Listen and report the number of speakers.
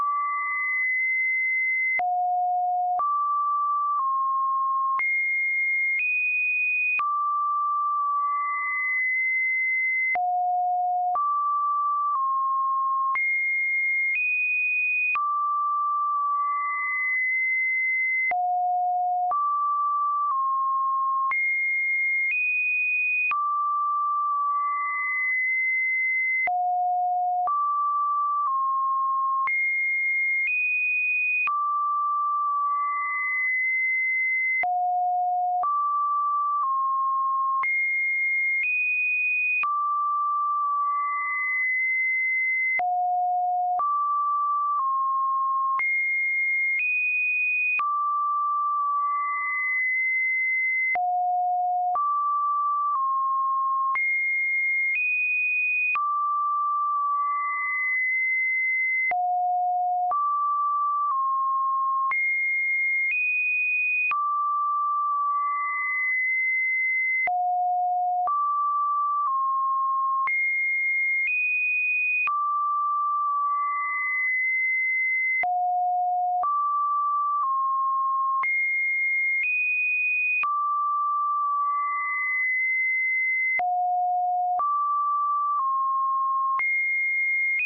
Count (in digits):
0